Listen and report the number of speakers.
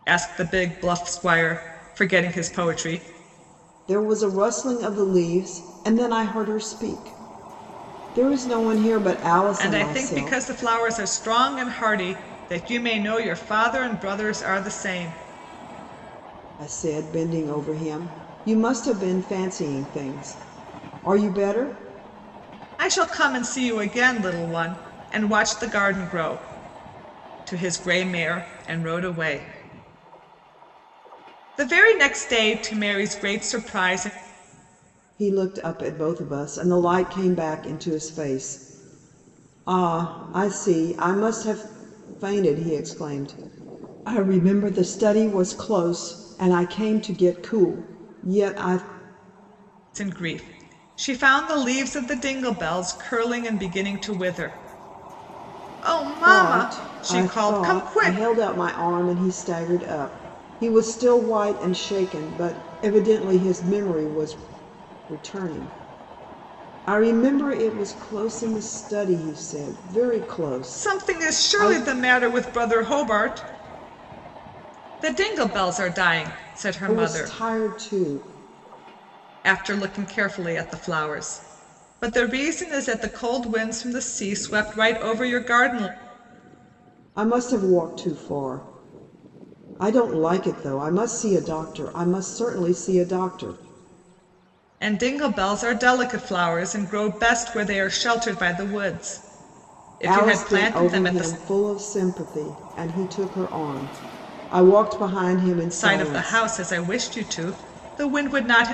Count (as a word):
two